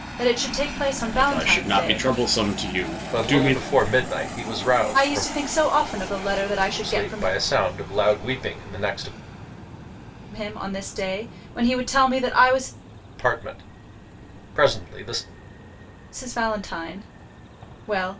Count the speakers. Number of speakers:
three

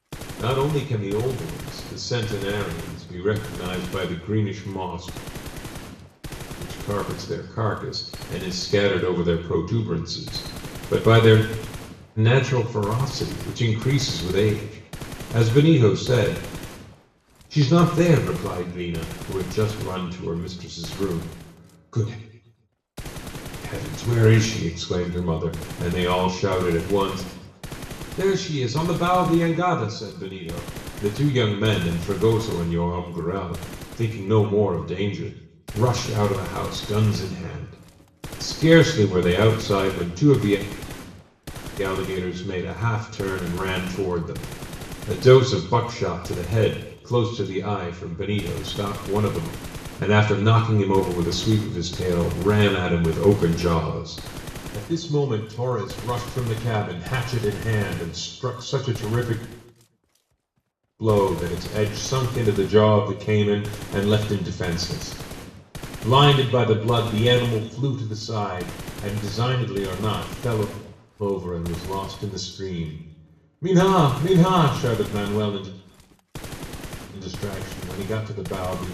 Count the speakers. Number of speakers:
one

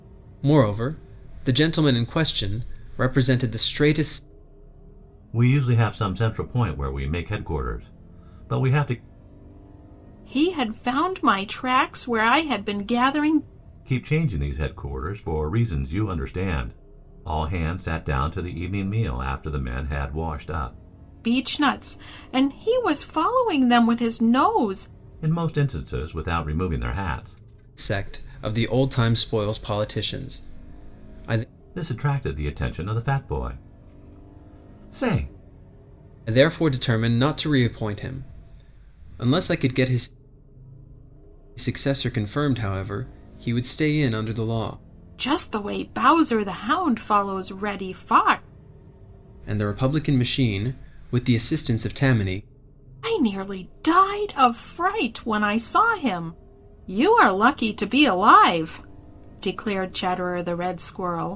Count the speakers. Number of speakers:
three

